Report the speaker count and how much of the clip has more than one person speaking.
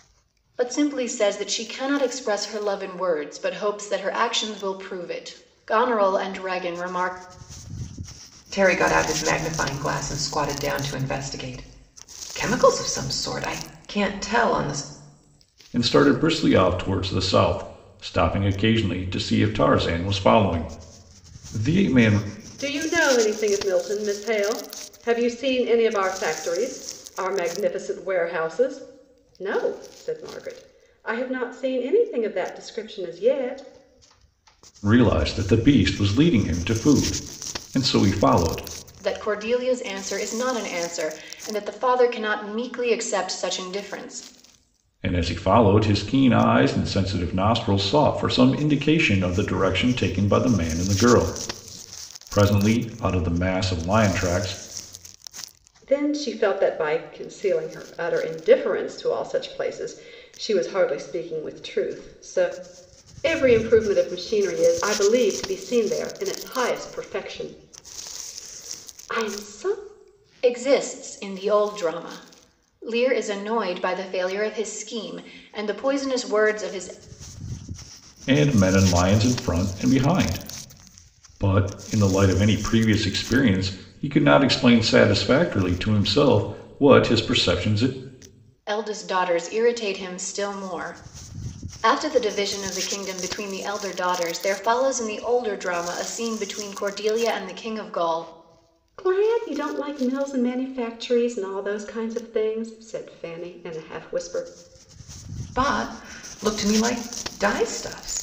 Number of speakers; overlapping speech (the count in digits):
4, no overlap